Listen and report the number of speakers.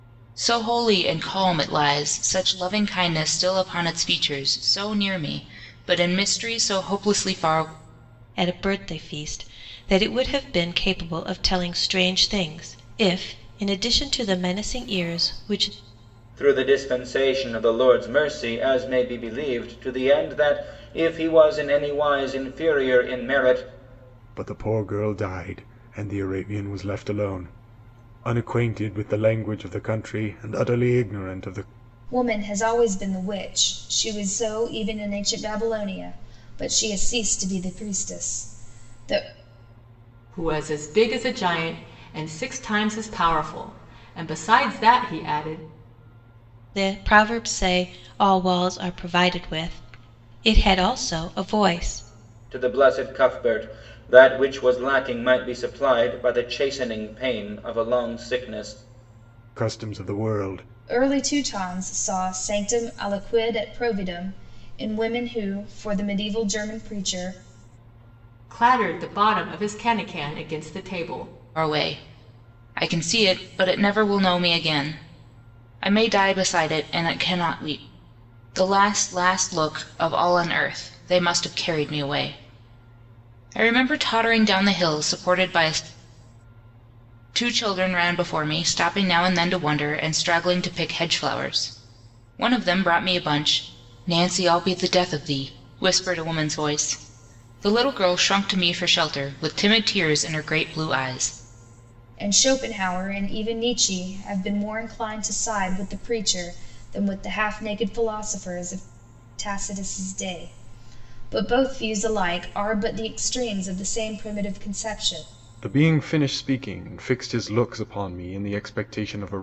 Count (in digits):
6